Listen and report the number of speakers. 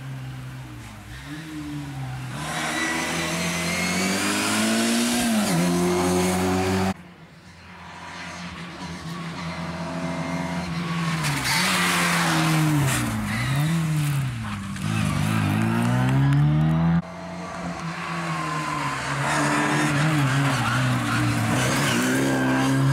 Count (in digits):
0